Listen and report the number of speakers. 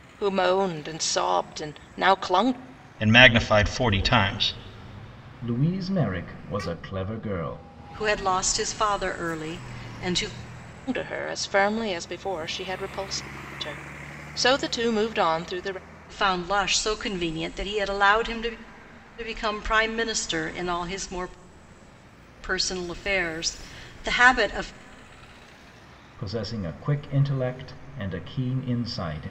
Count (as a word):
four